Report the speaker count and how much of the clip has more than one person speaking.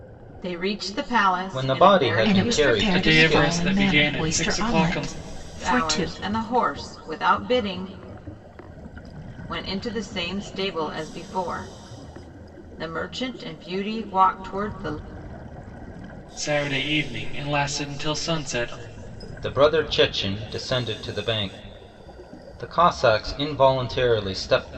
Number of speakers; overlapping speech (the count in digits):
4, about 17%